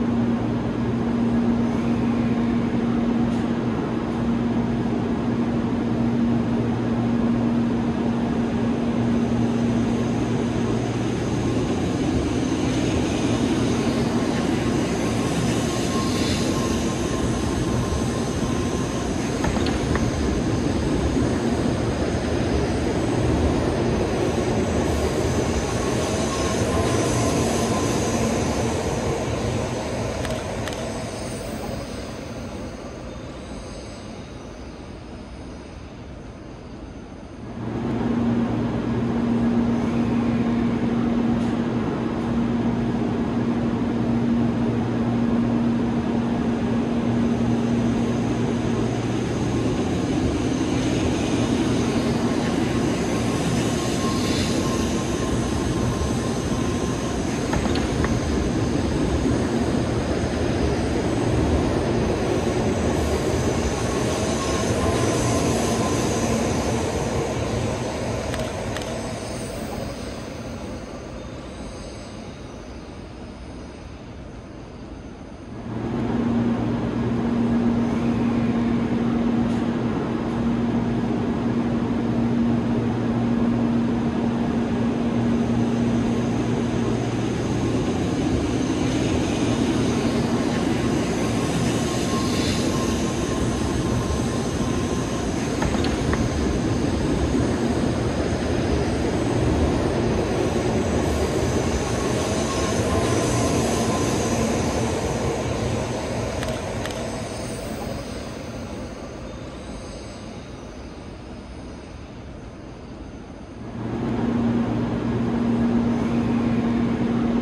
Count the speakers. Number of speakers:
0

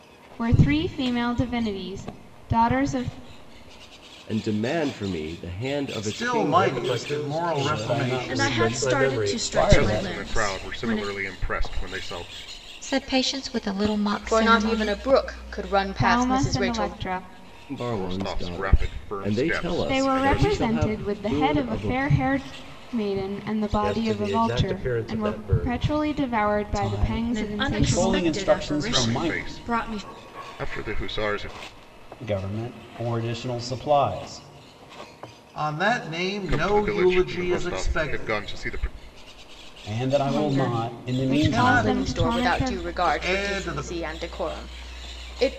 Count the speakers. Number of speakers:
9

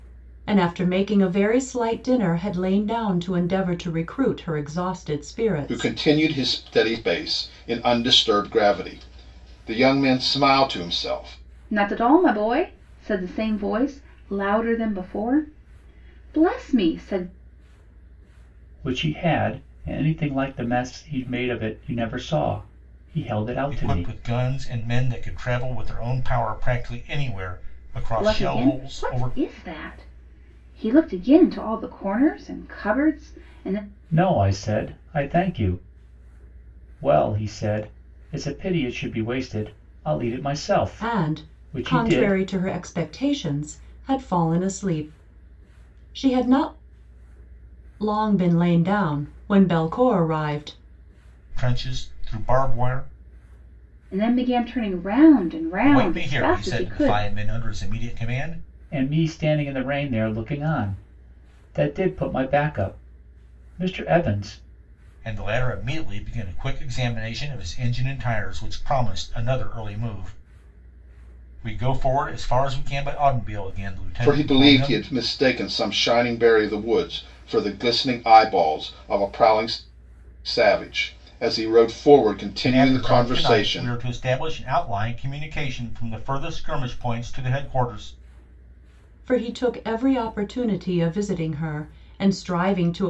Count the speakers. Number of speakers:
5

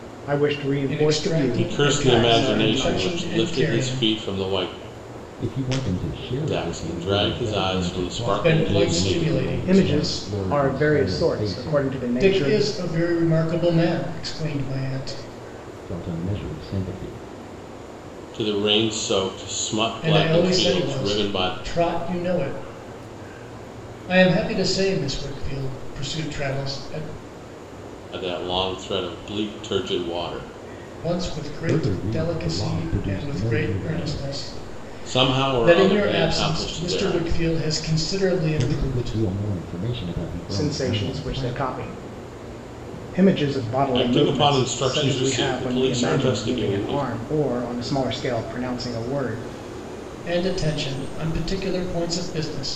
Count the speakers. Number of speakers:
4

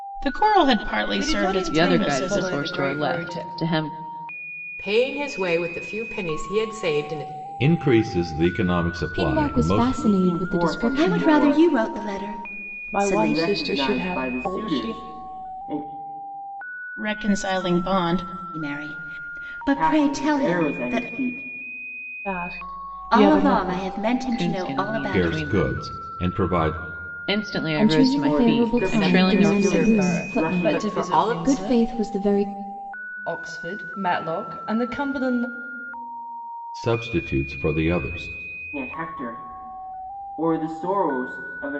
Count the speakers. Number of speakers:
9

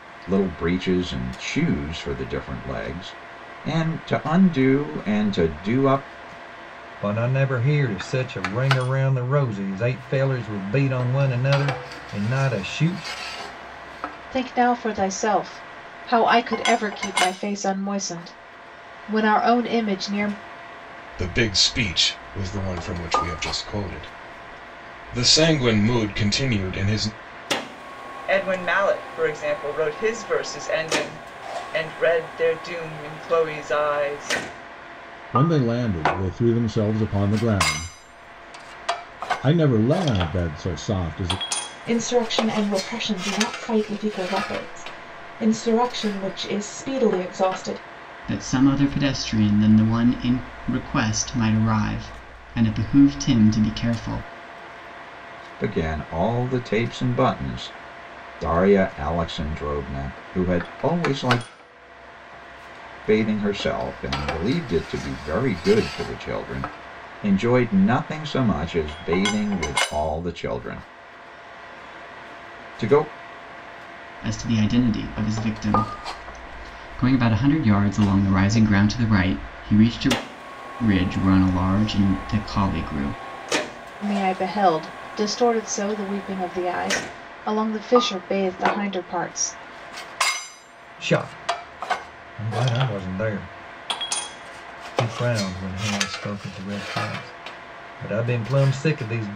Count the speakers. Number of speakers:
8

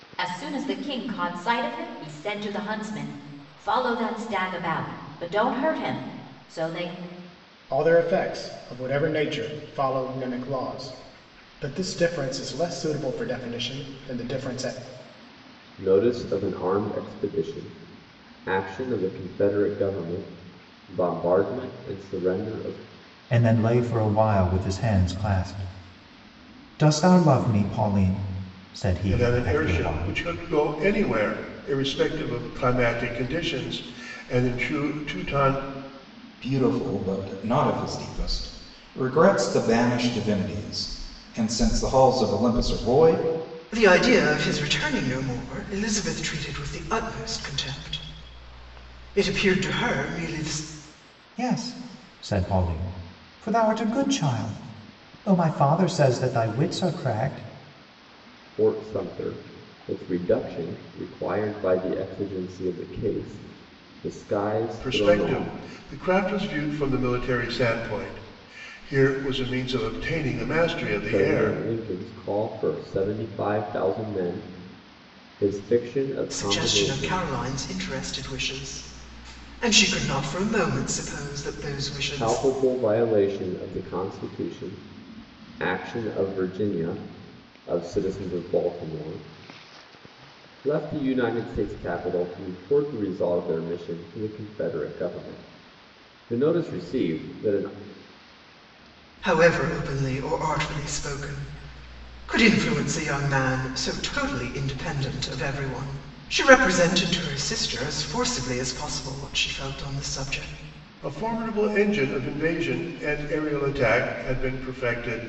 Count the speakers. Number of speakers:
7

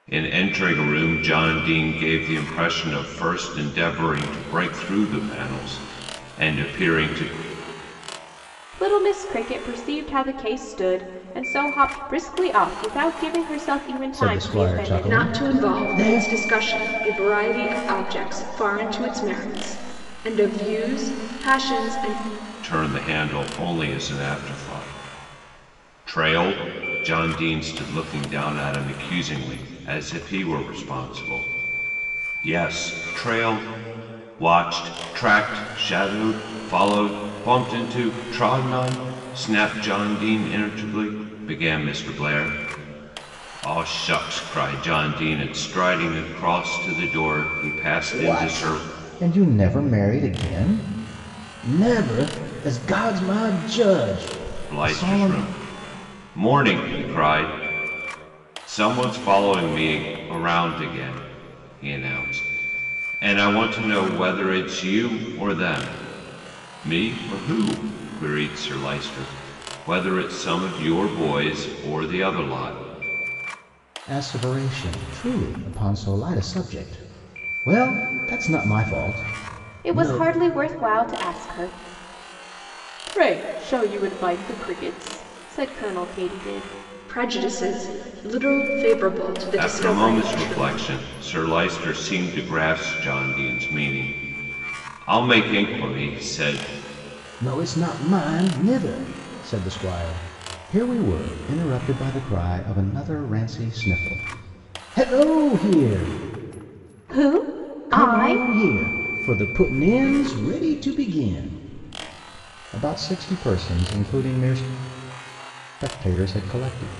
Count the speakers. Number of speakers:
4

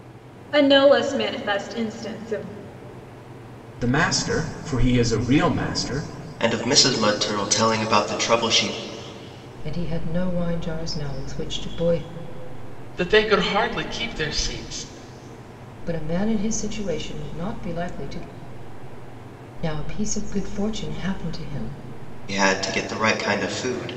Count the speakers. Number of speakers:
5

